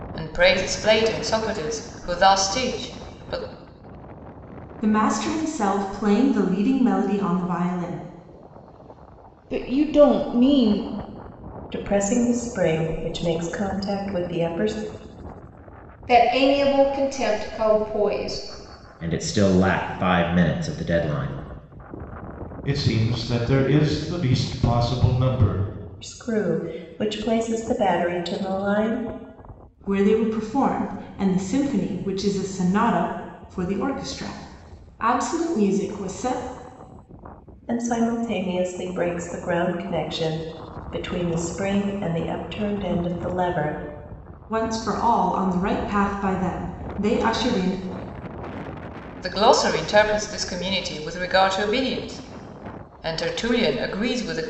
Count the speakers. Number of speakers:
7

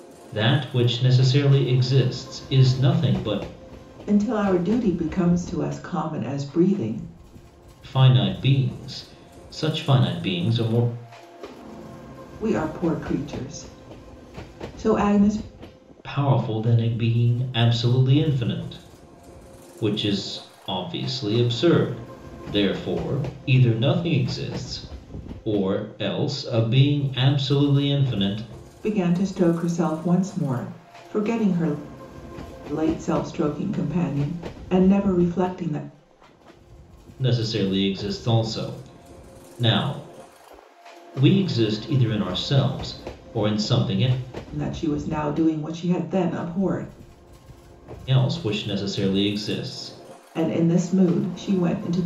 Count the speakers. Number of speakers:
2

